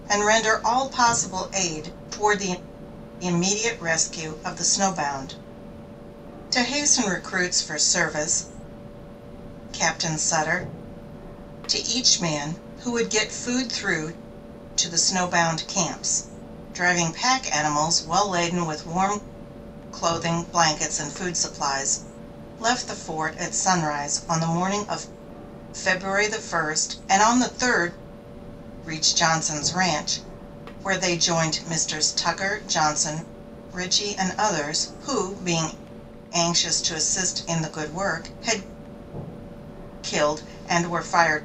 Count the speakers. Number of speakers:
1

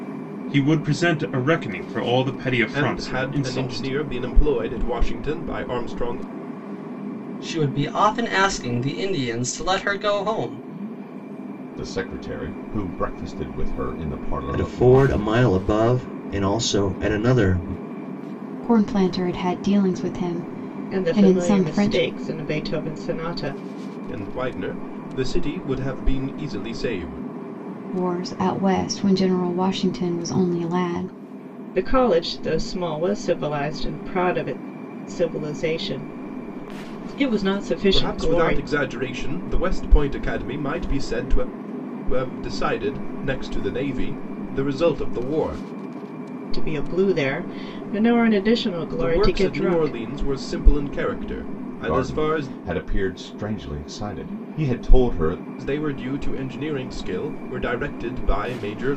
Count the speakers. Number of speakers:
7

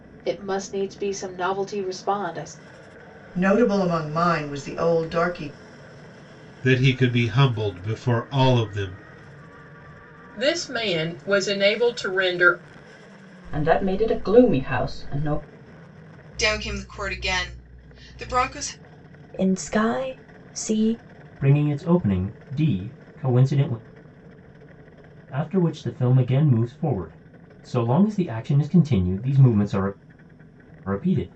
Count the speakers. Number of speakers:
8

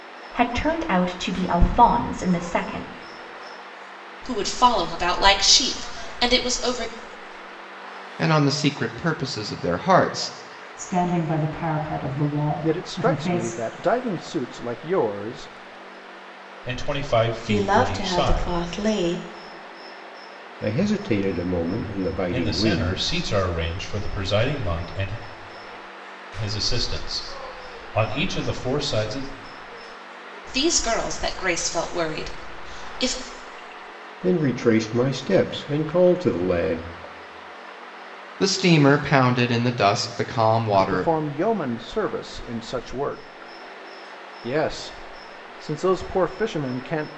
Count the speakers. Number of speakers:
8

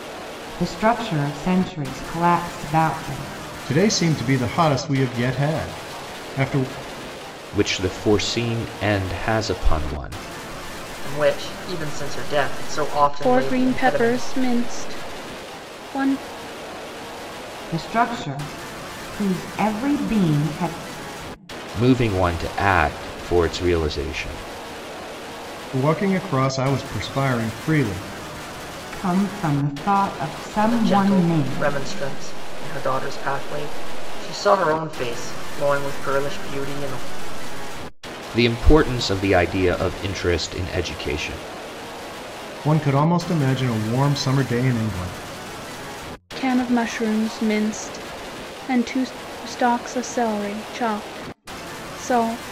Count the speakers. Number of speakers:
5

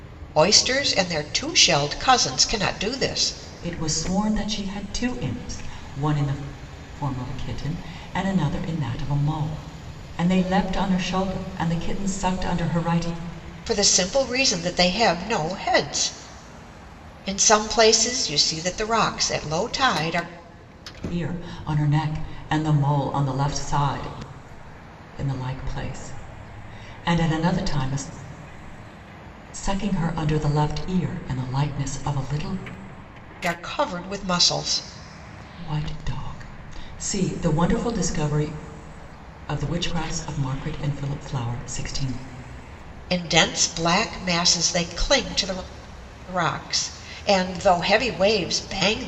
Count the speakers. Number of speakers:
2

